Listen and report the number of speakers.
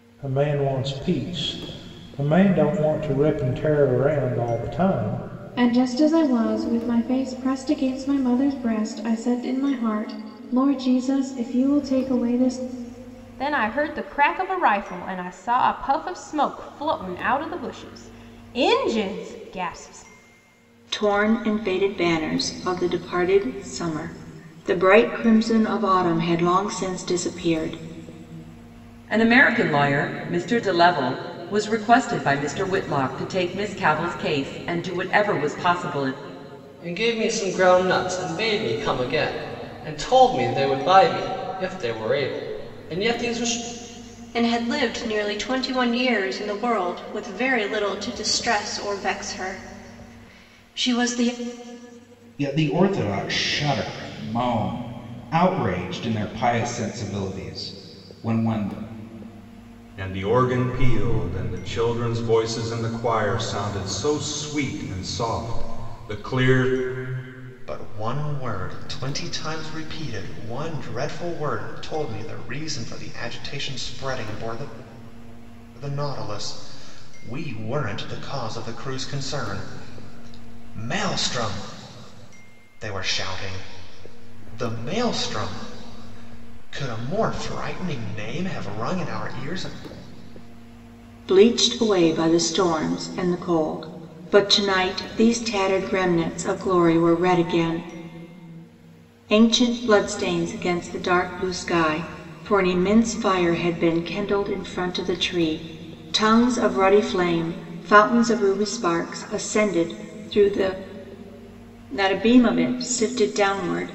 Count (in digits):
10